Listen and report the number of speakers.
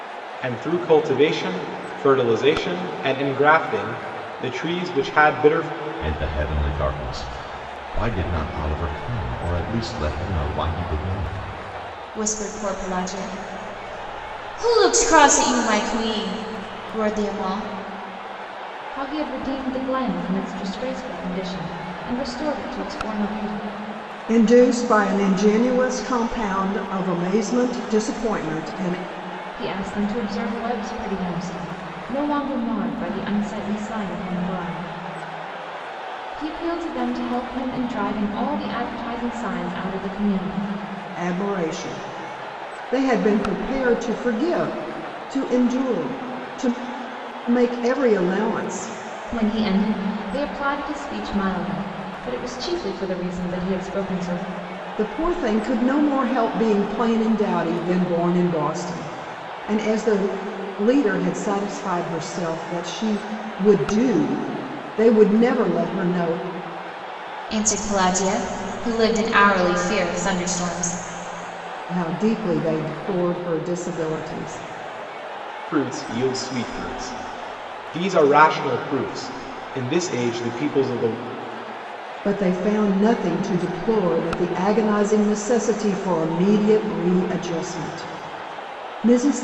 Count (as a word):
five